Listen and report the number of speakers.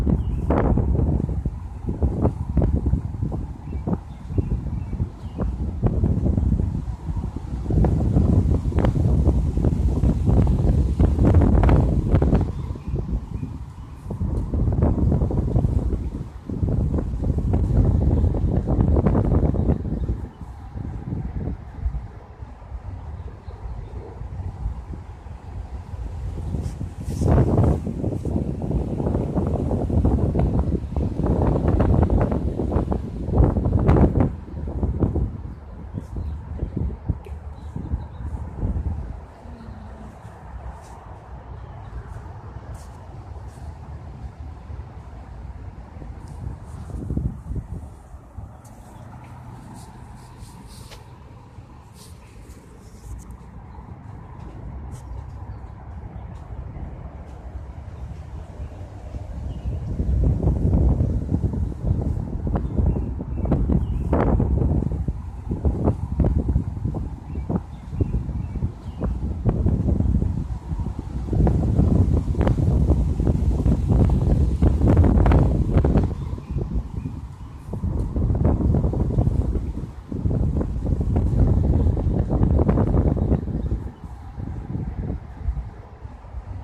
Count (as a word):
zero